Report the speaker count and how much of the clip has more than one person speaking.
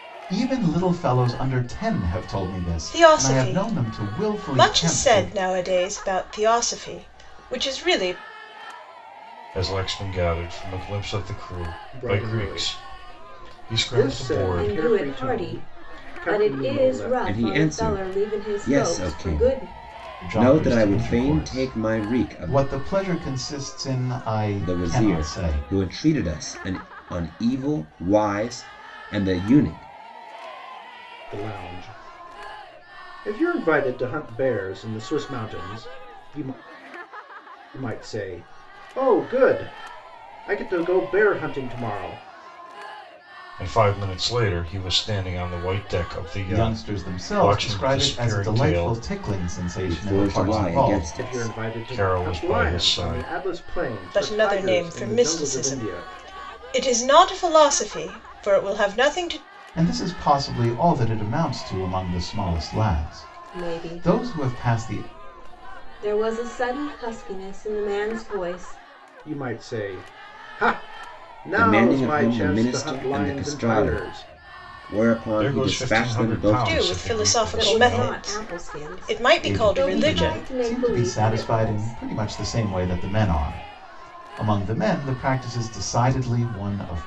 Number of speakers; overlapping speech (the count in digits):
6, about 38%